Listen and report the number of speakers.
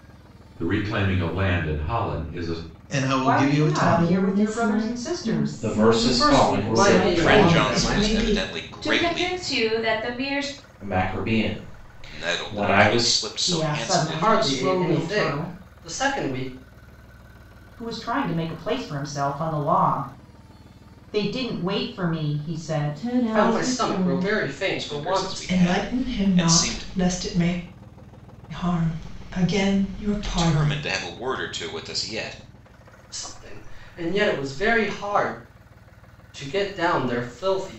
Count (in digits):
9